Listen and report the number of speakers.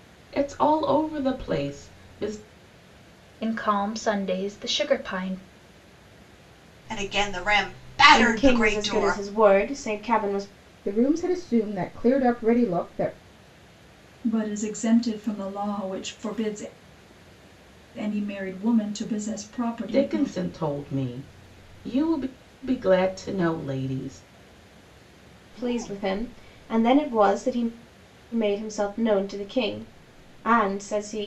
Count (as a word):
six